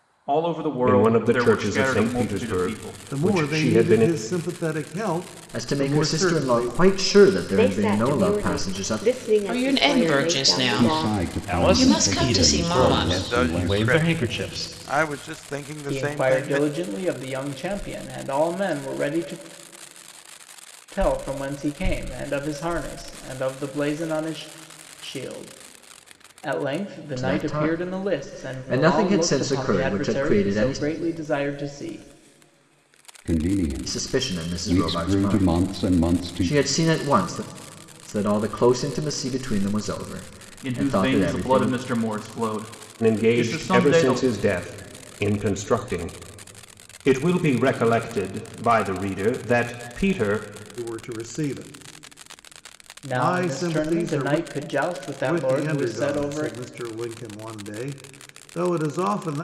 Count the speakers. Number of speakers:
ten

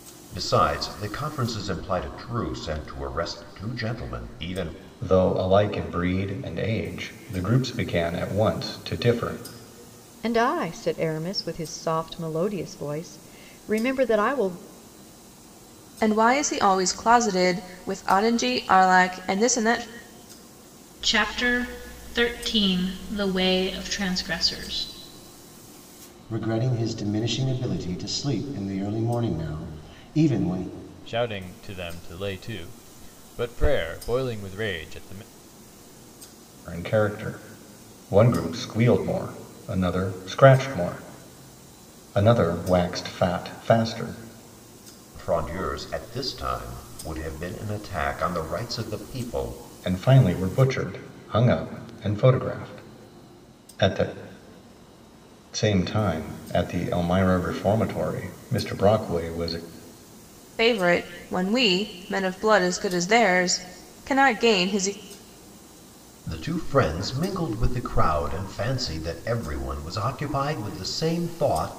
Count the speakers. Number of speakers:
seven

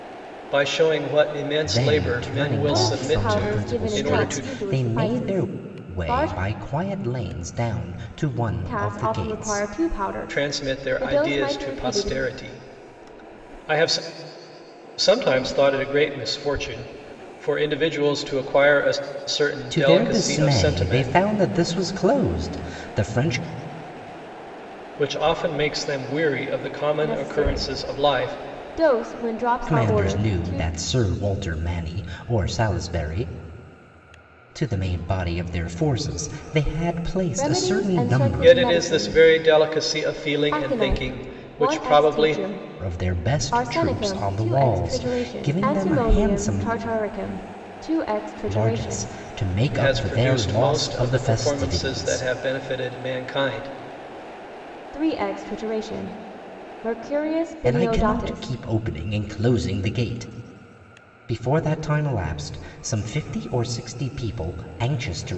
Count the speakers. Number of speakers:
three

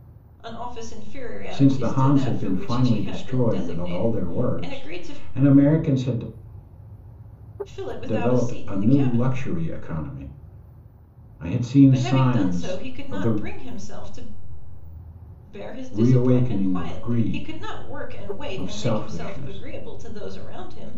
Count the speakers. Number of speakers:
two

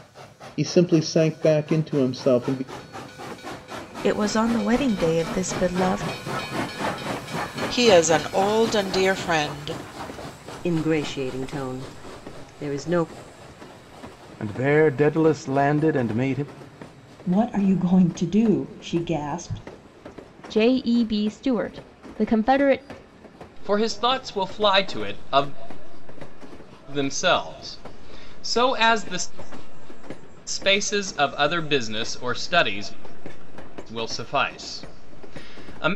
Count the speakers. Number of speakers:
eight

